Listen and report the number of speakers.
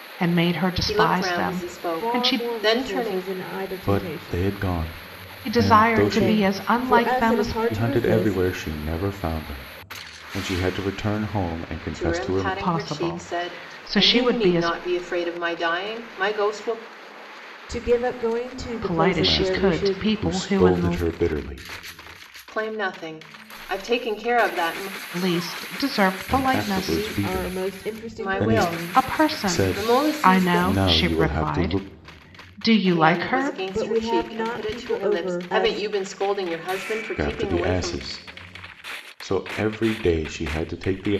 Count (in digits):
4